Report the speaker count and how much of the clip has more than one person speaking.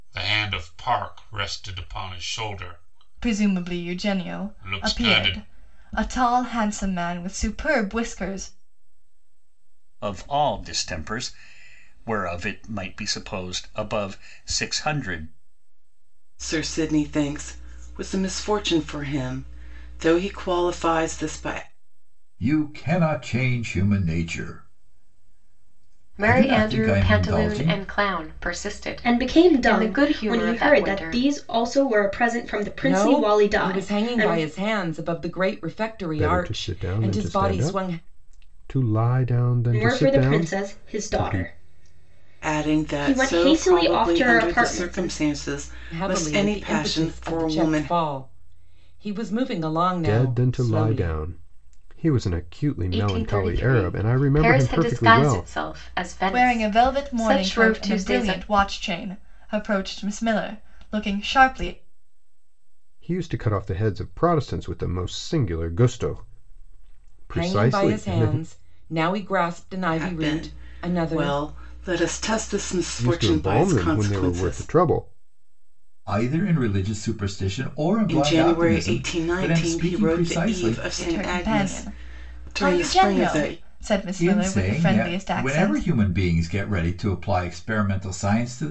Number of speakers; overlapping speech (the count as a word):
nine, about 38%